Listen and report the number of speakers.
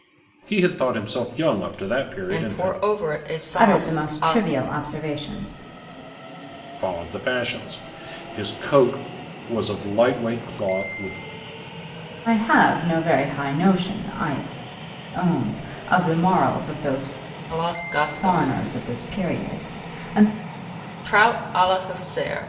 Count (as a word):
three